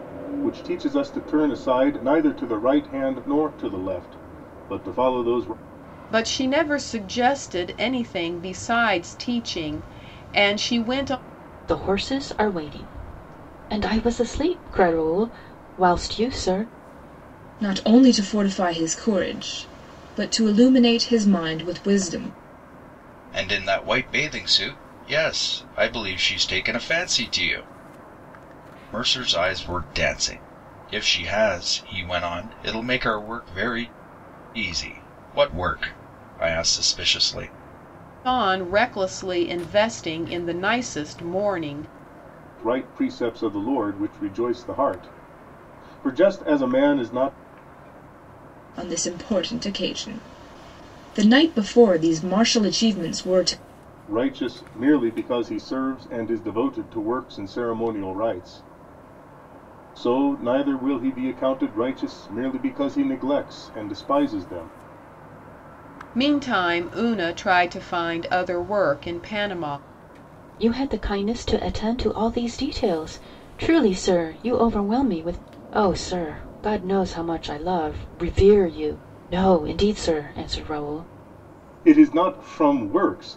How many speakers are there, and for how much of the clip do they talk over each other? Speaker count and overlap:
five, no overlap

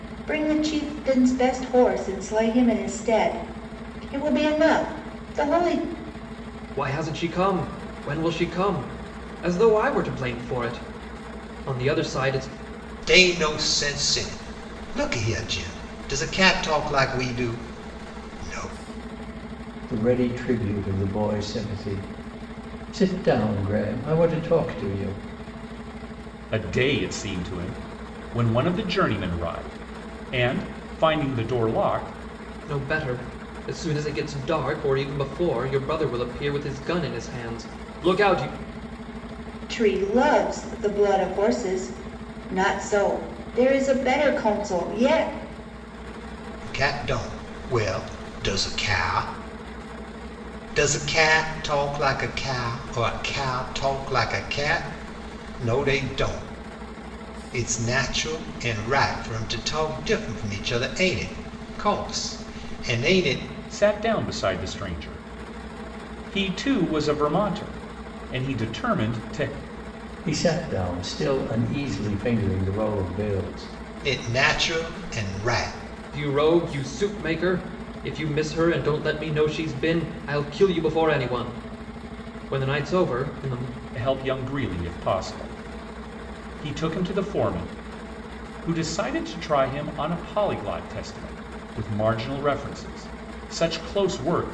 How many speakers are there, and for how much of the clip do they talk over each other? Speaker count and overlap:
five, no overlap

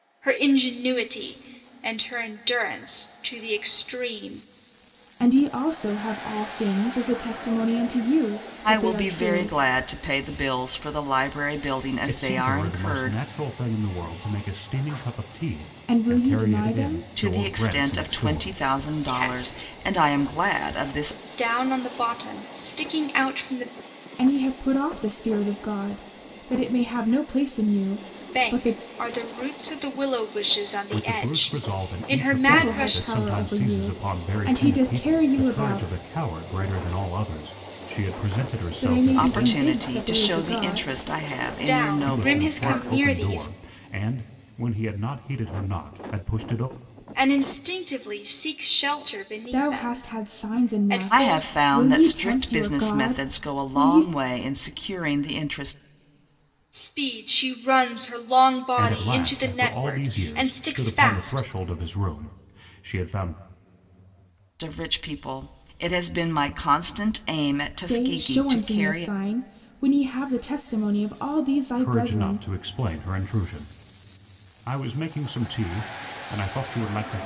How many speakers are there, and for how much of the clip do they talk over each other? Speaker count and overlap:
four, about 34%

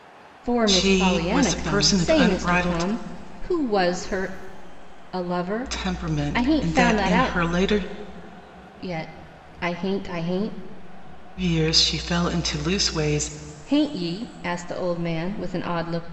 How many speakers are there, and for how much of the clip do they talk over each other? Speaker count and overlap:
two, about 25%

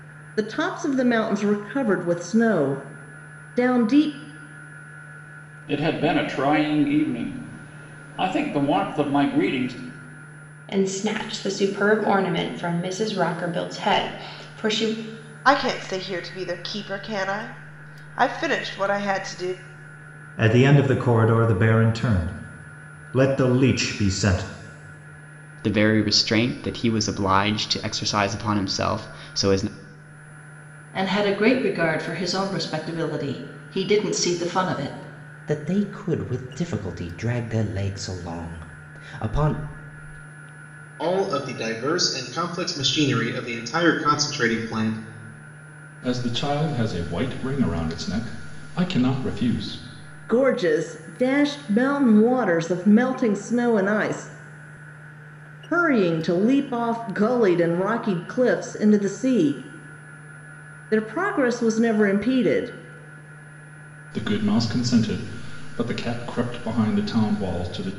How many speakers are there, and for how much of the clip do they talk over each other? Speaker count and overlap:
ten, no overlap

